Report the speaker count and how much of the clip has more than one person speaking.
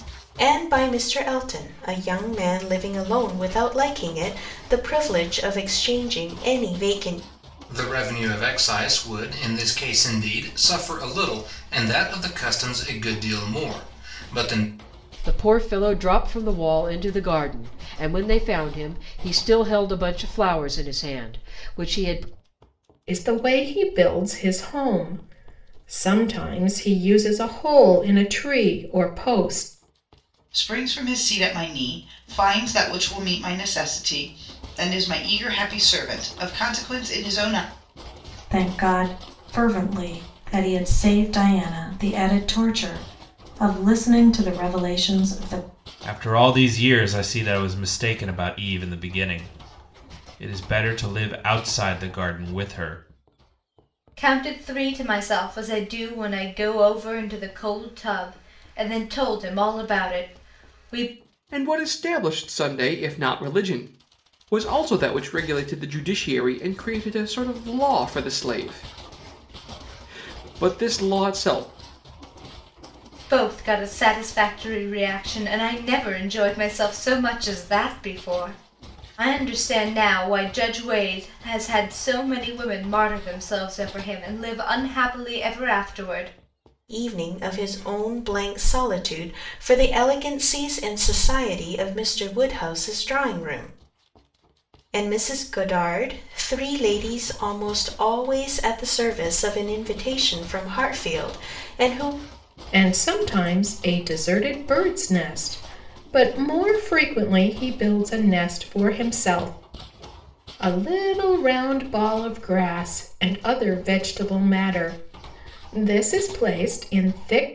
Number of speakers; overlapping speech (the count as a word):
nine, no overlap